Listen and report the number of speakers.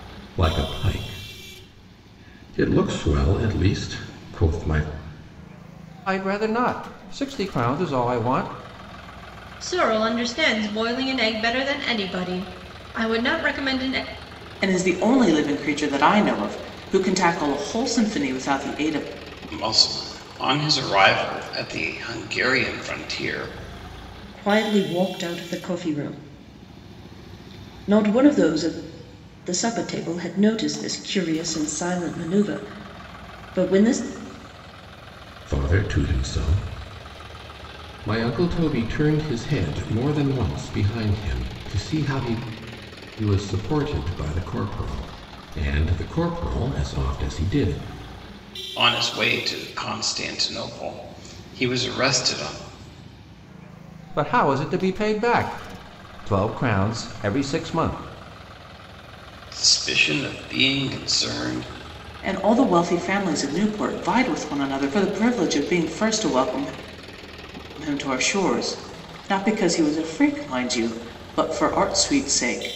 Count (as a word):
six